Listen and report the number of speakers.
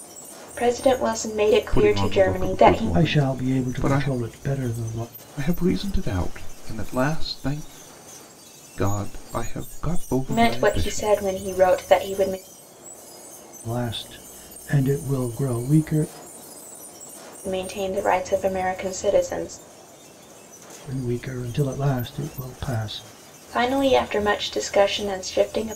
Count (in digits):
3